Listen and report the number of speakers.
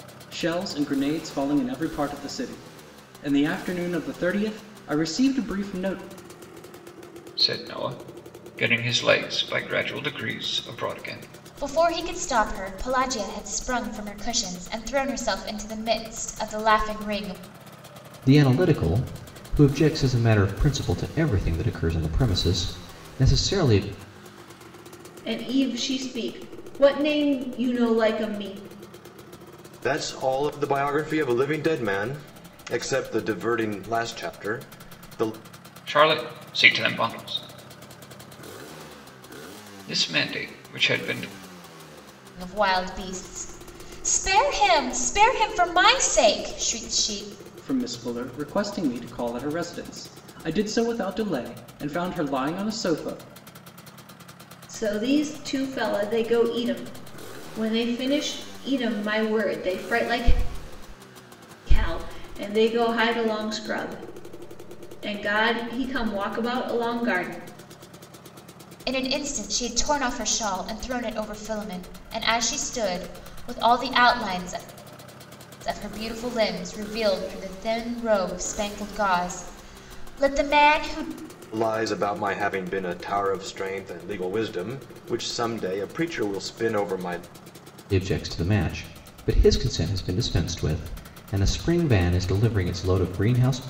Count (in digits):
6